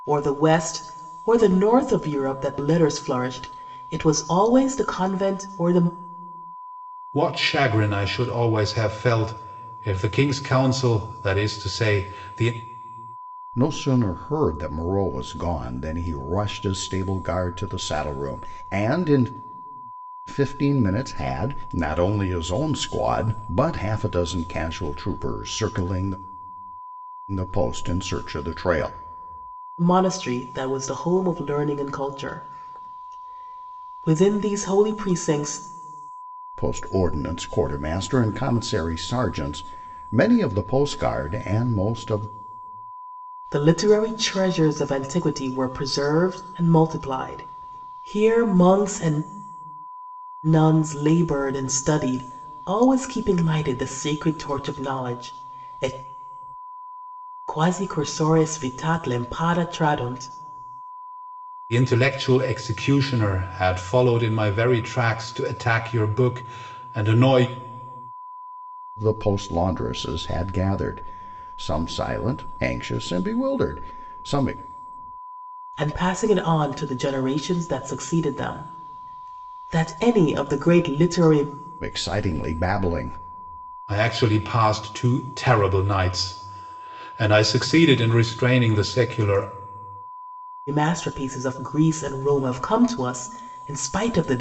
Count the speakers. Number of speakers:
three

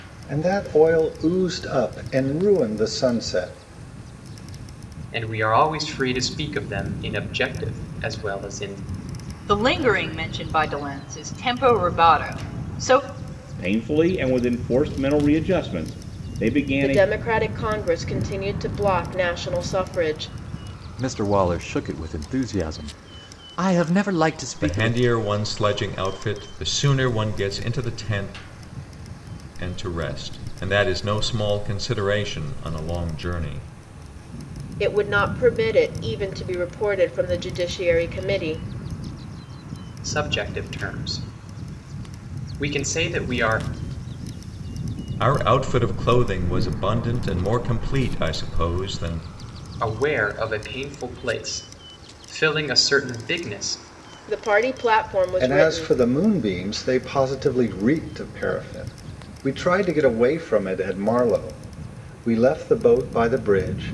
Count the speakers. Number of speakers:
seven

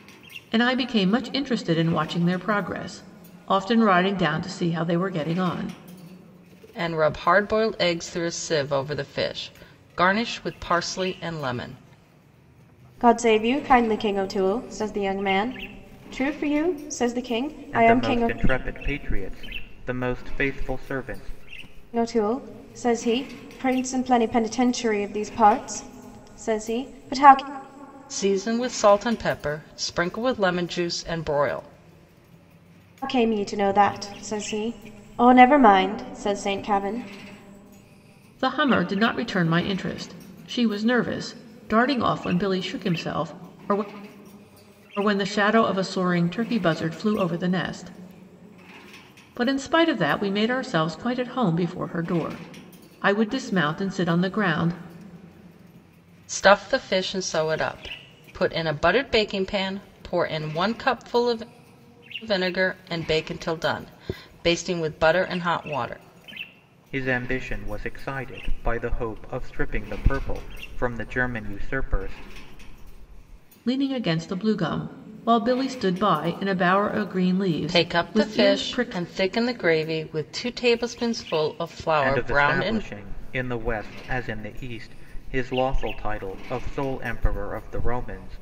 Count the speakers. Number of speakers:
four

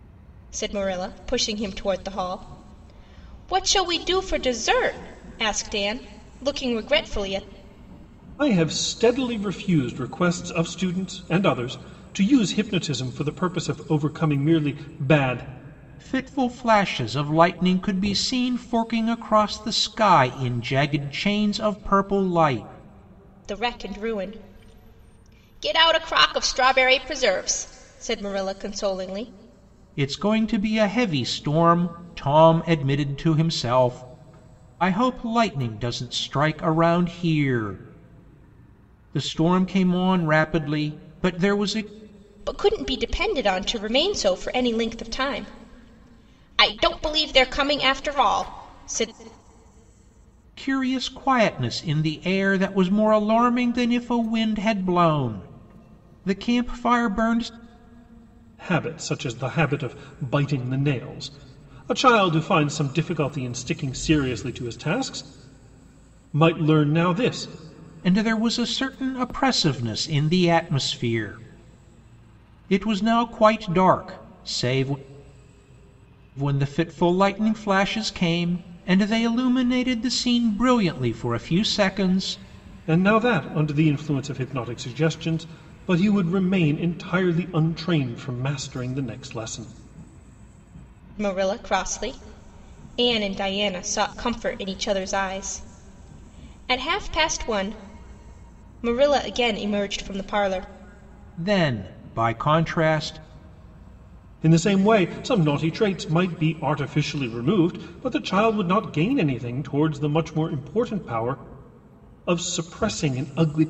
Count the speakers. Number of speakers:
three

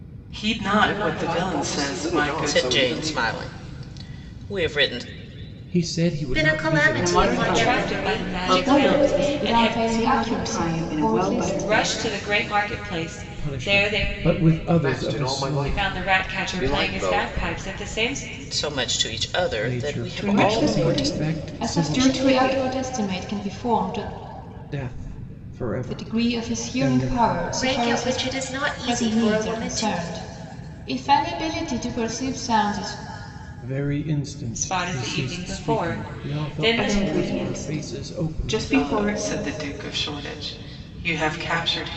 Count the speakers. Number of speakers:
eight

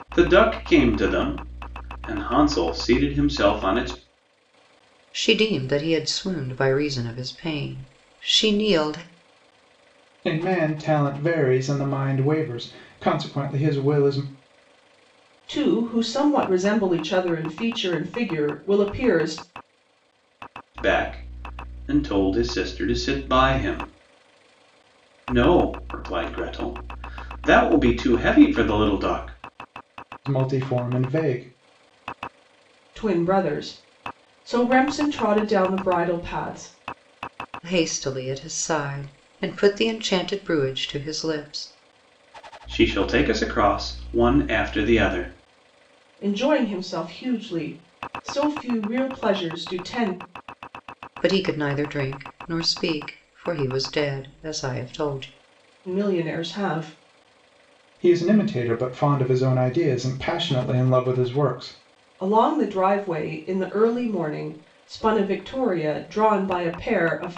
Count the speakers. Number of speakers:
four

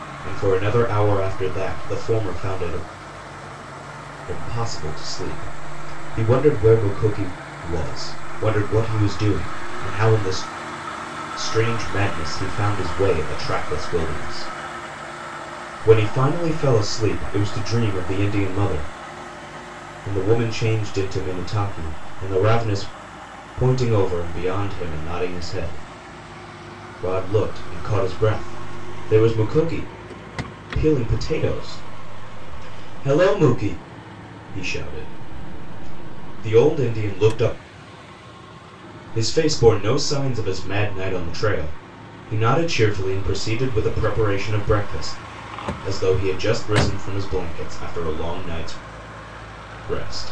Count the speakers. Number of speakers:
one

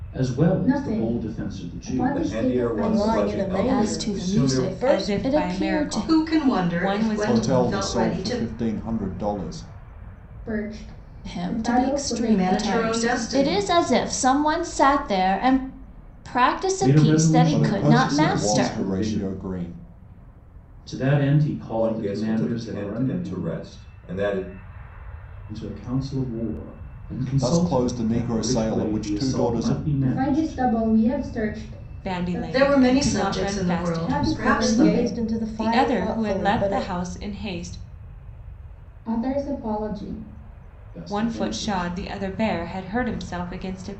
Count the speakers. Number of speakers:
eight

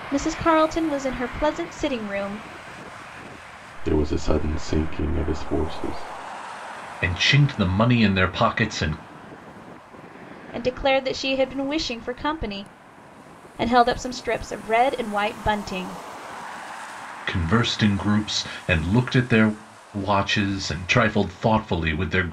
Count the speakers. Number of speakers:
three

